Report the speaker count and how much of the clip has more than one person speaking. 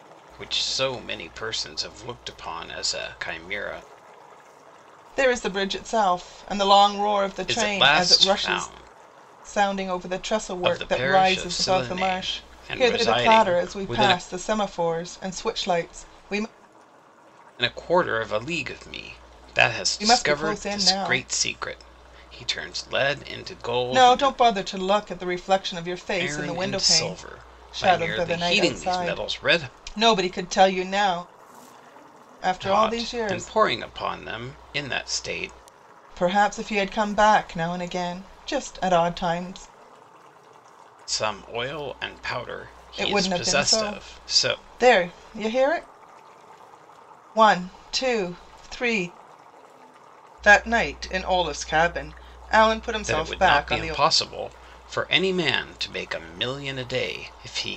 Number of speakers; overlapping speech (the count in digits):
2, about 23%